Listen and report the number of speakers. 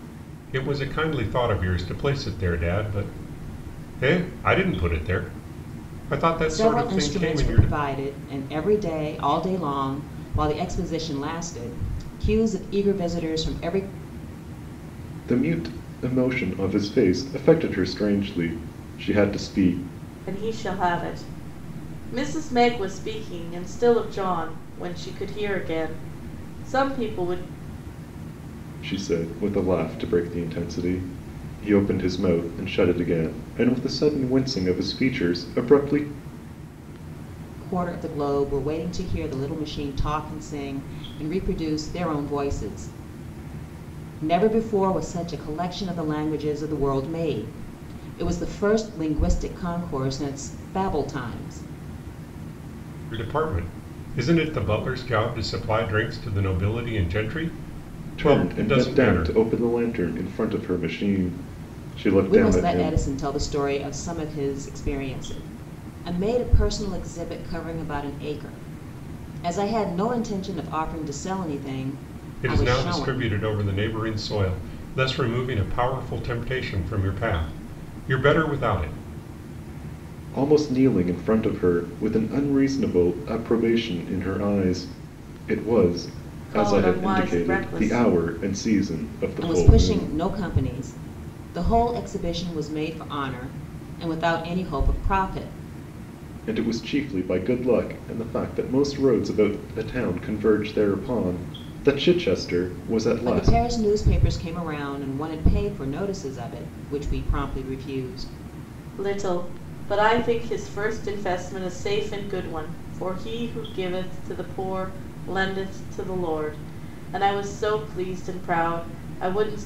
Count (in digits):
4